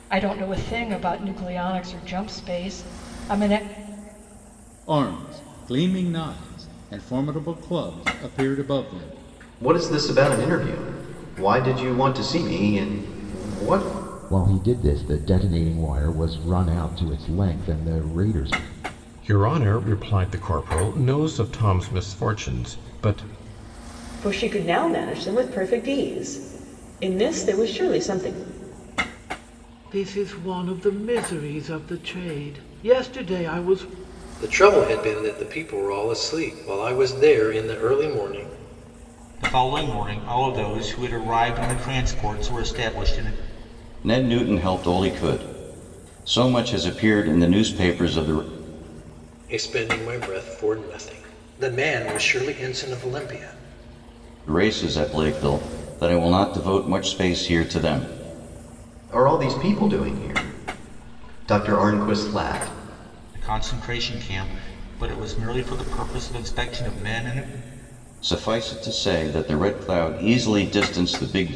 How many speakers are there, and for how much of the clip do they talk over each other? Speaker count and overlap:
10, no overlap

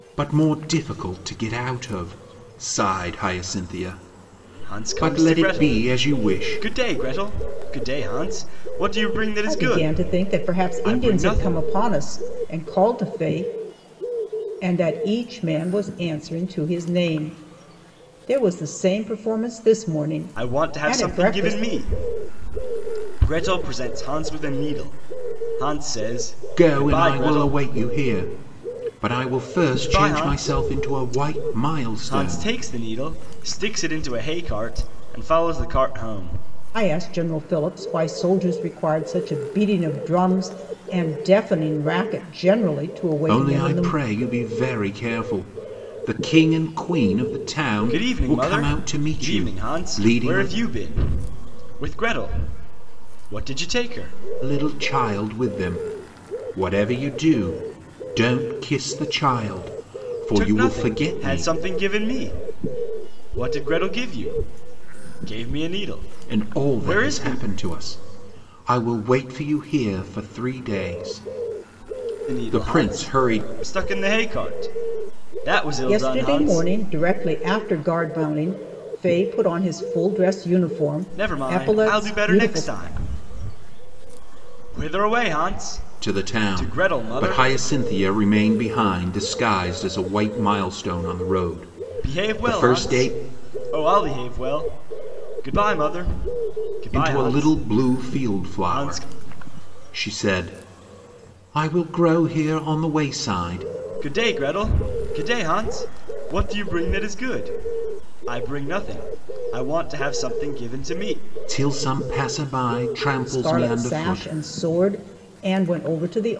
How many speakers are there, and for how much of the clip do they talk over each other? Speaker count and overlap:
3, about 21%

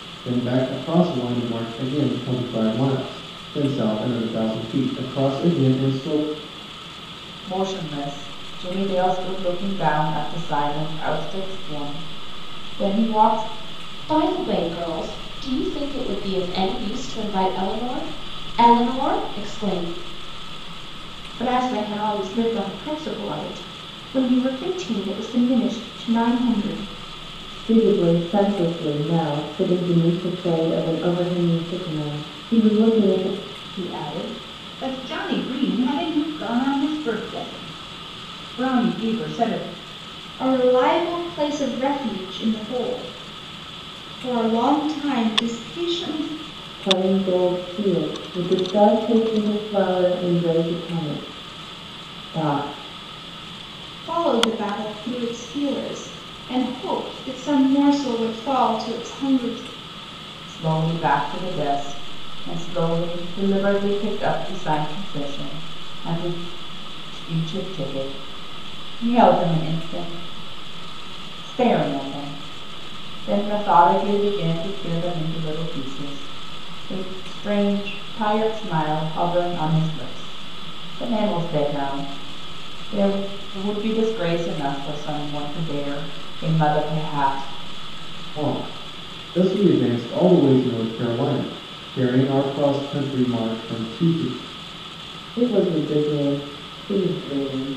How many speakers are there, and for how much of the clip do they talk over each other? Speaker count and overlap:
7, no overlap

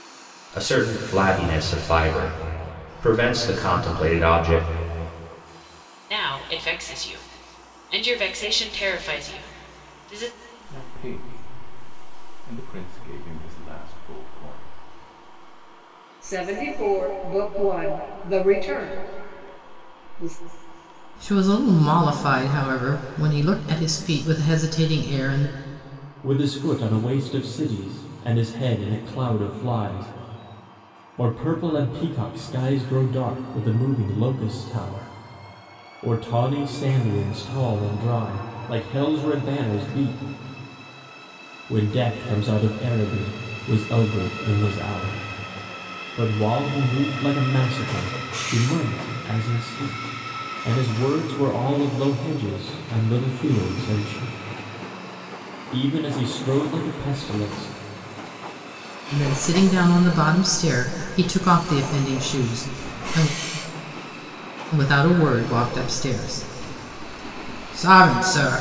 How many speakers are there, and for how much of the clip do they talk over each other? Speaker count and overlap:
6, no overlap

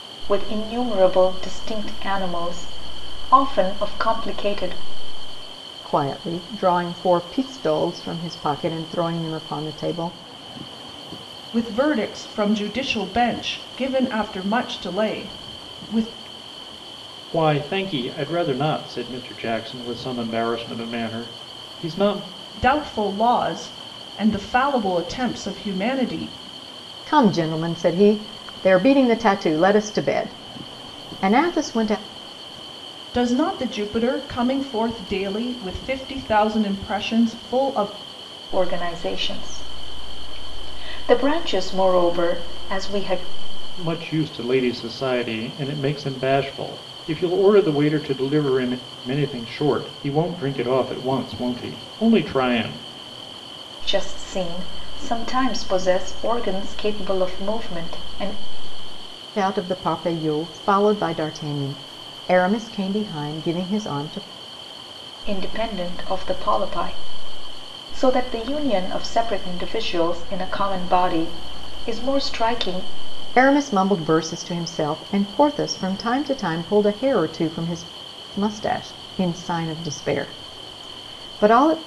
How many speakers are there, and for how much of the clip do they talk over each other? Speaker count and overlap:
4, no overlap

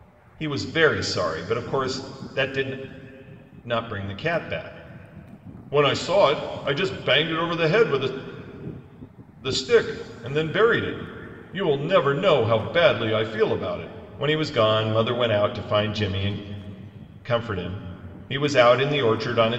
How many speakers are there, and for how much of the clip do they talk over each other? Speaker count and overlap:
1, no overlap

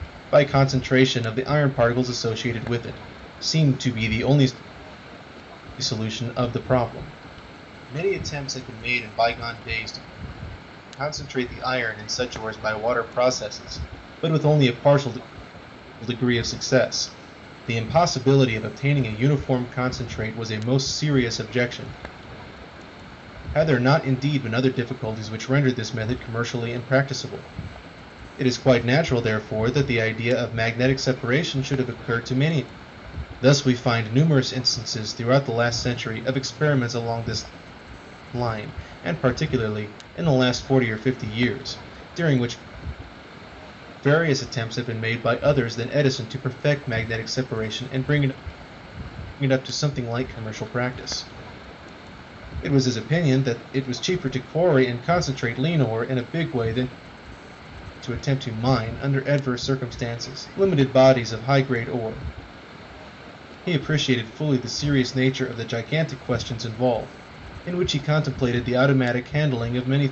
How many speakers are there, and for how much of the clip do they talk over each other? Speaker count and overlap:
1, no overlap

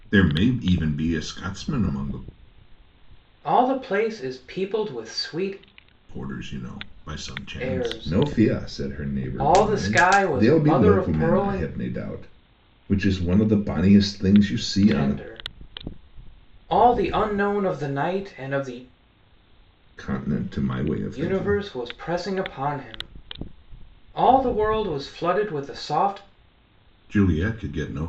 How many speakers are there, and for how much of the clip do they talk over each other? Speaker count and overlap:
2, about 12%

